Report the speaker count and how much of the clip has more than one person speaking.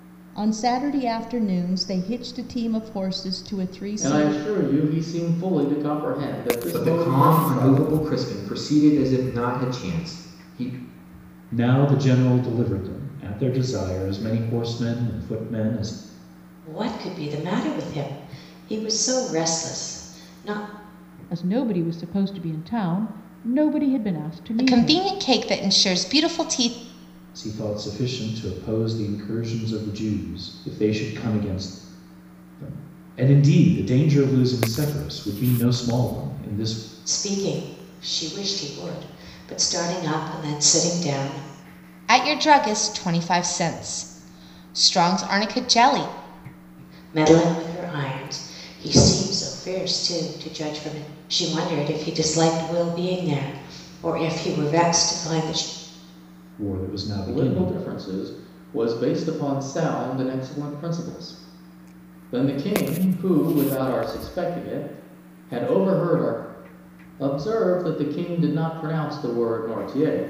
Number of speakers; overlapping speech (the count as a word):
seven, about 4%